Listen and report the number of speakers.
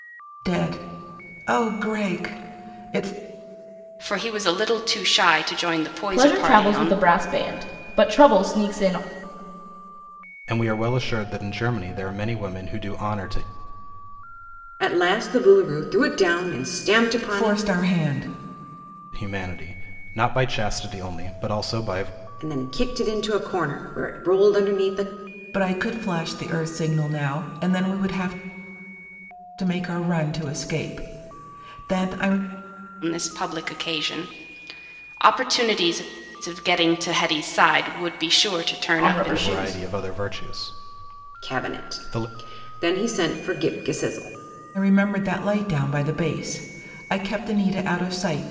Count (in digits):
5